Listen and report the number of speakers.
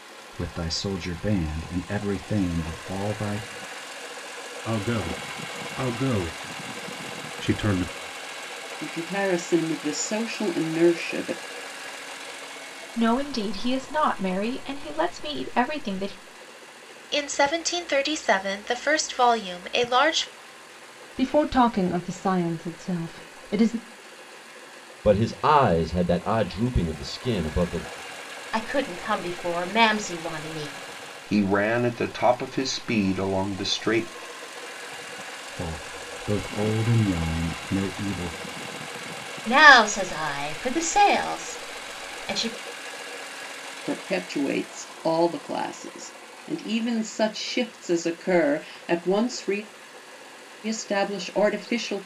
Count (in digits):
9